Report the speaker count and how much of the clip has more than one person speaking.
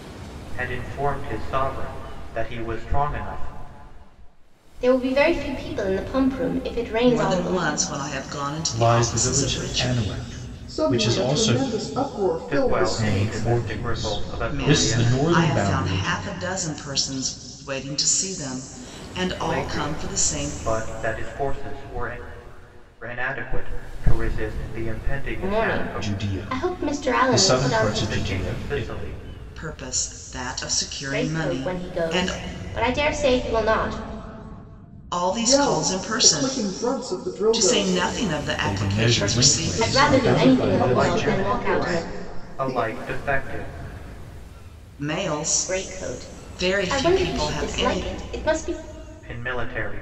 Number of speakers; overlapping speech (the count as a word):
five, about 42%